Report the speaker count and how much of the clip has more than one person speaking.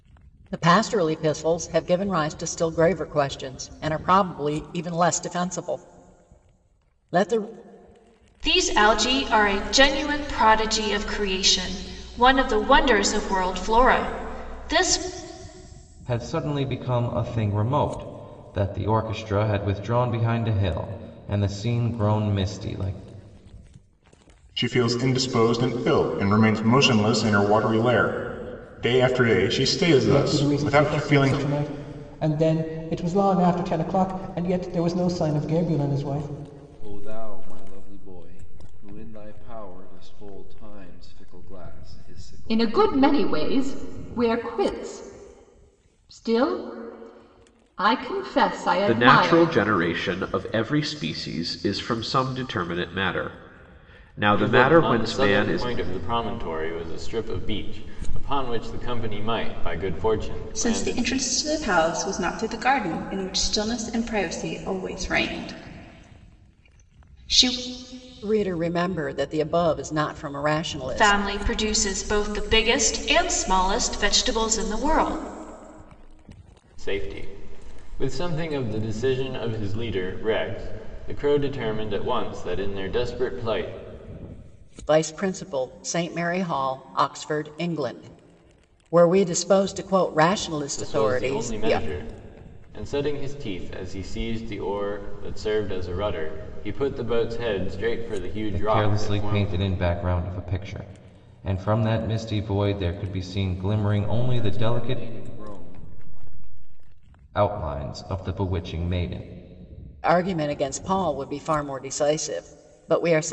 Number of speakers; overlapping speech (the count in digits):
10, about 7%